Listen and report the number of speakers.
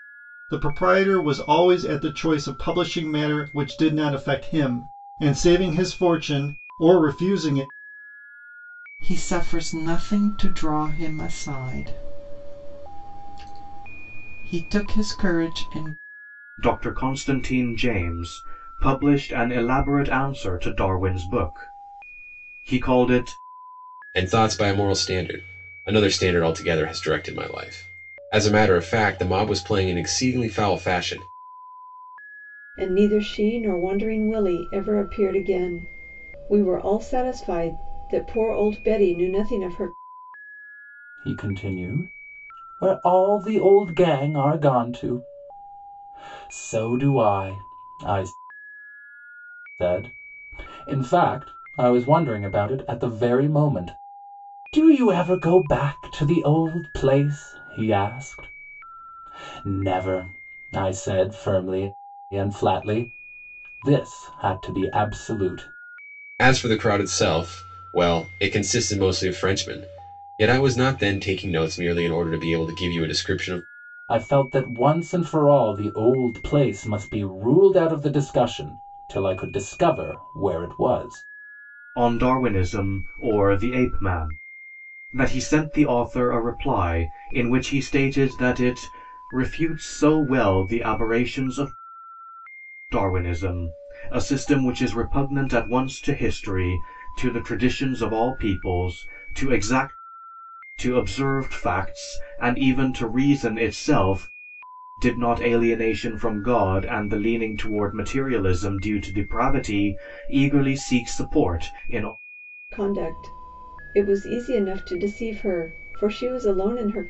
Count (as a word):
six